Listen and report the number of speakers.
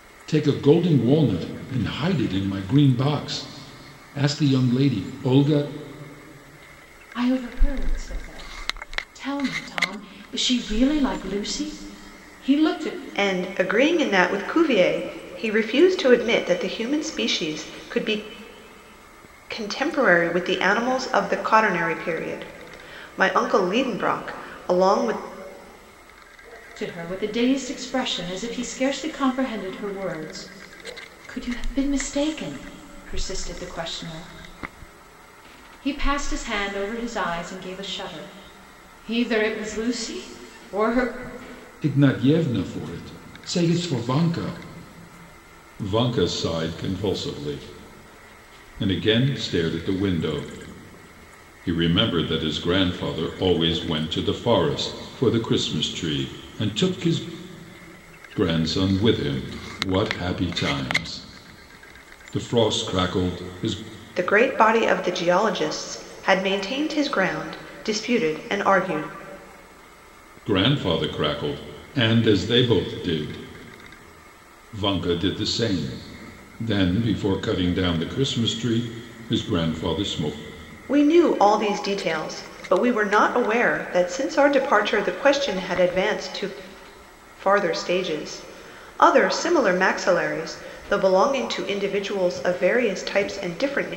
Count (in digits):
3